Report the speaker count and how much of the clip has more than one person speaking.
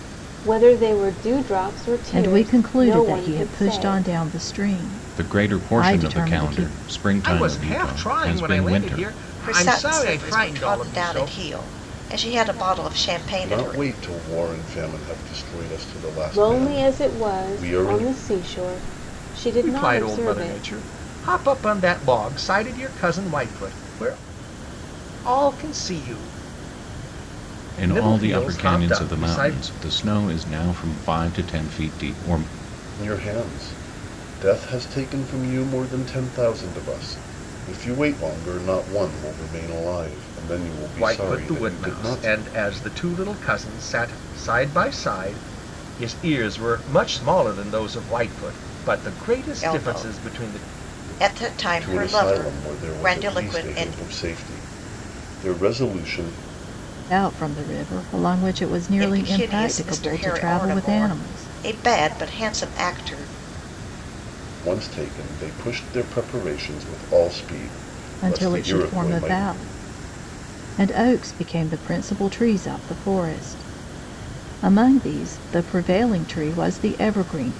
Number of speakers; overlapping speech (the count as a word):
six, about 27%